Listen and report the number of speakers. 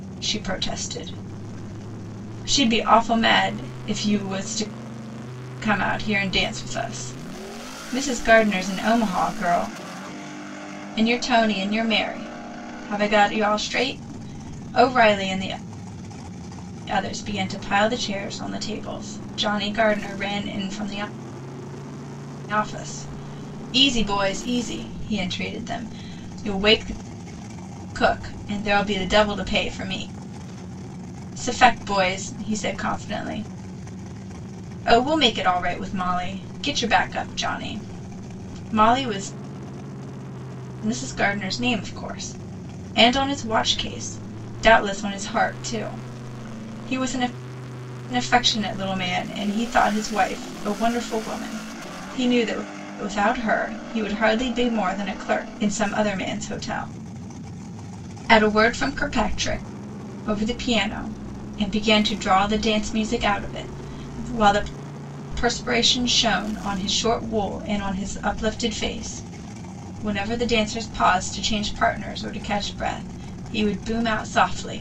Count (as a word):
one